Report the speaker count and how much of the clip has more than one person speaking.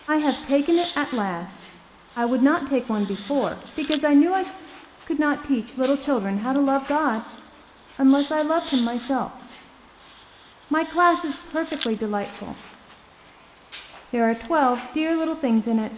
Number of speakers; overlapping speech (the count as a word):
one, no overlap